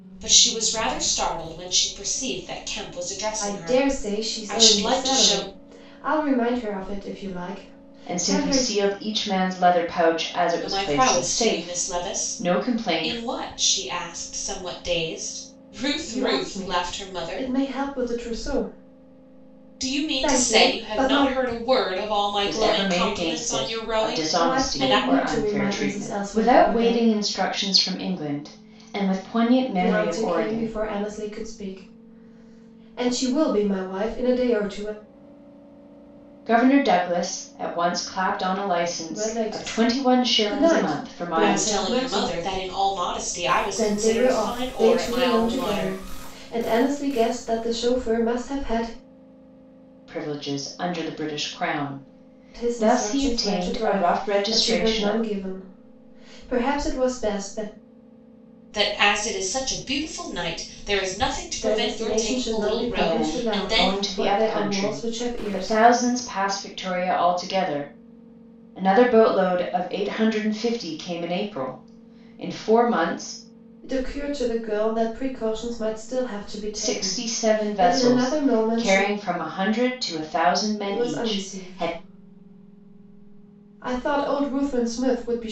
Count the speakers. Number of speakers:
3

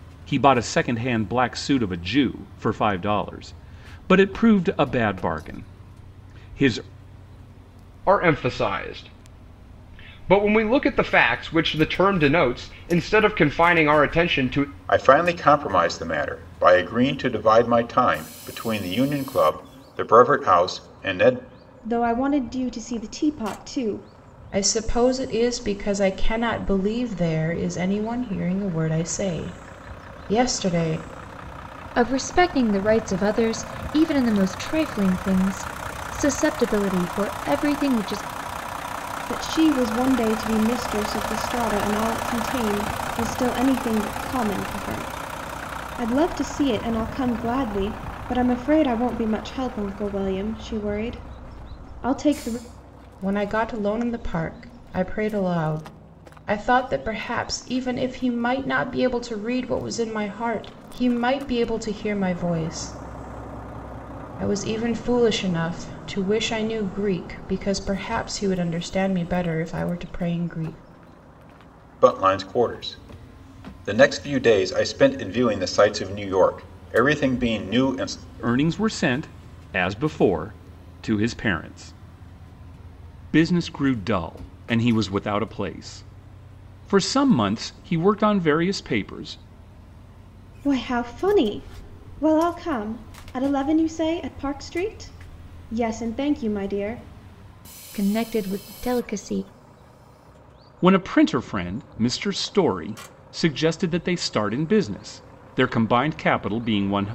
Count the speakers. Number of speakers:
6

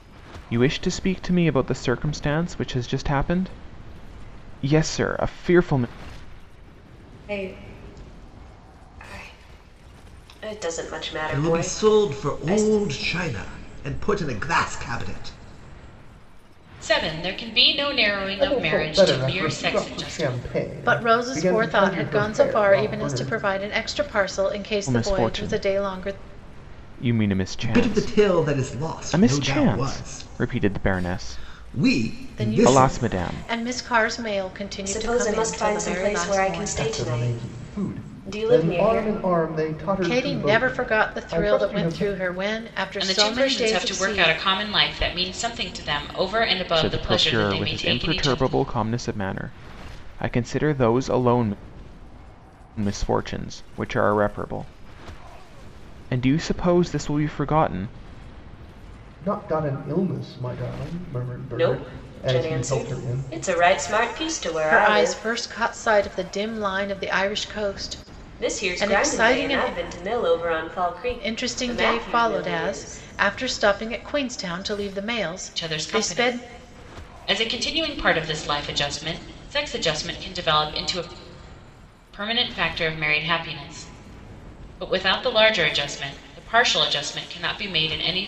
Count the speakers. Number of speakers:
6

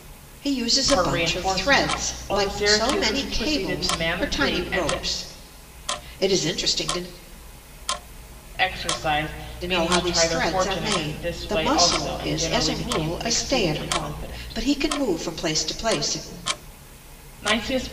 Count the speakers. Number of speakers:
2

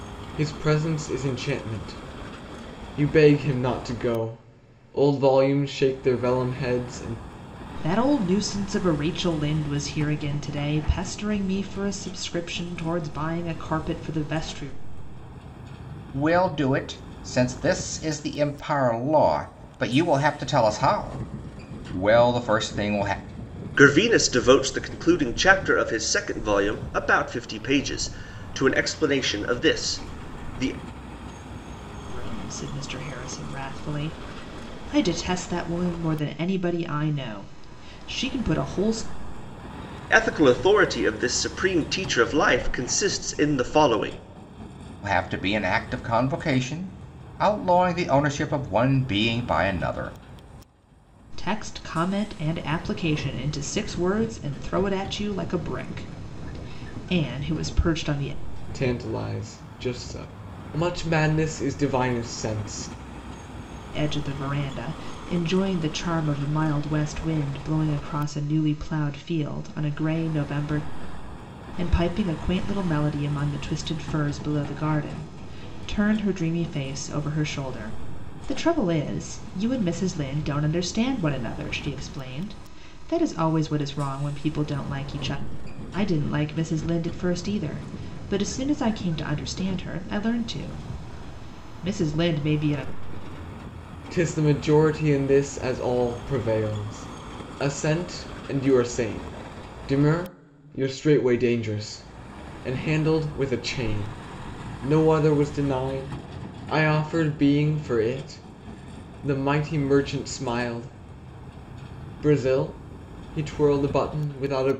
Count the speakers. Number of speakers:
4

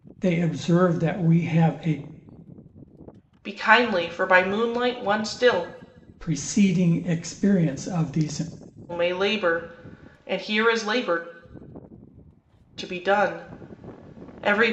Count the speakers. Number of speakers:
2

